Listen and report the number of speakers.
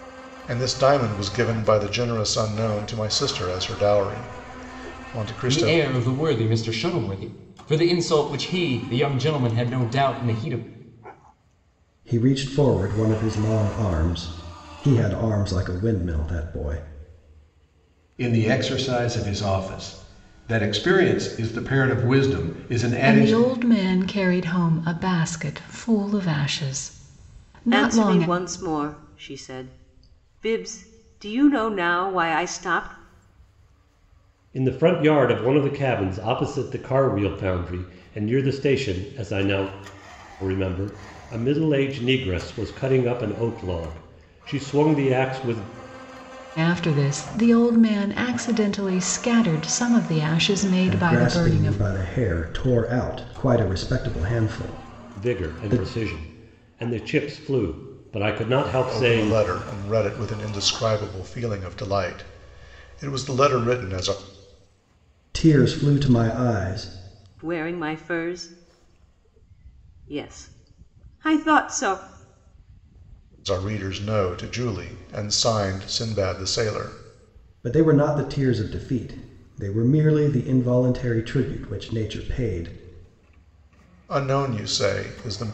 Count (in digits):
7